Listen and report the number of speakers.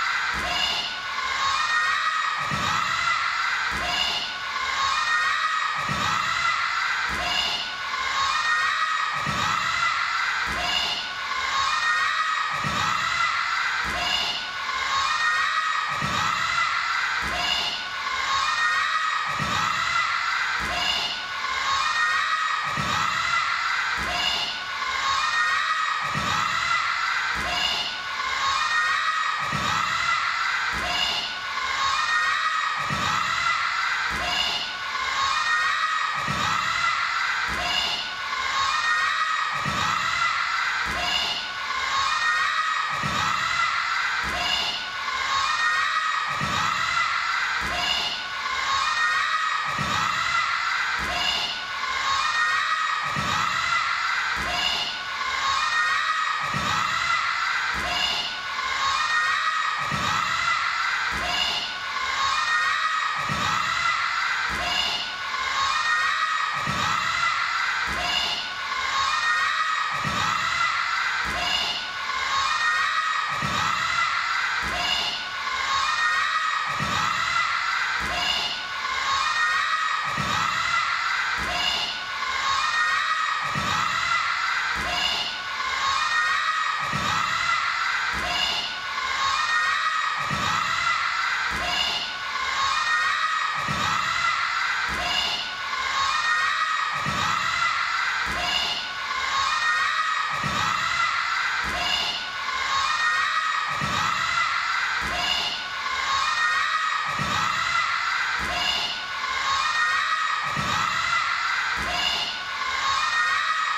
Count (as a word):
zero